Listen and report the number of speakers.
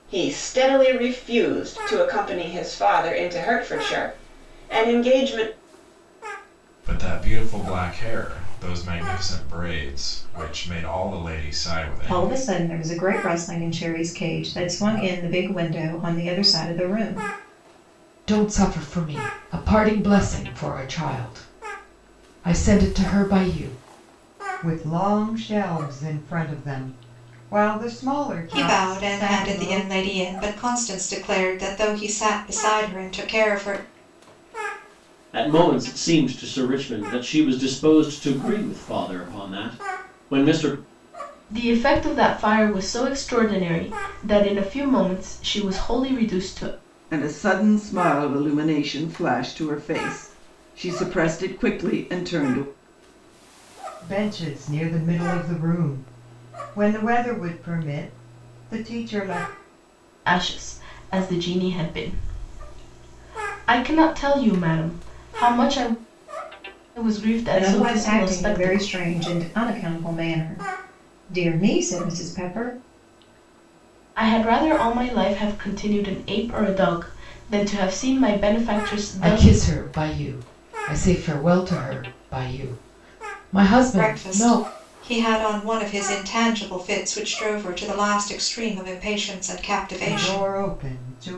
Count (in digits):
9